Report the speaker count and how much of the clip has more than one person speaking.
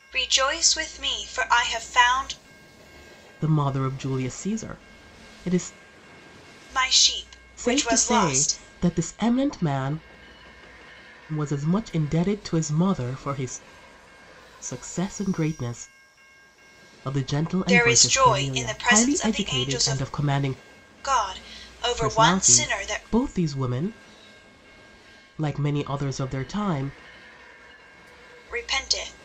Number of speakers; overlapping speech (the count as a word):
two, about 16%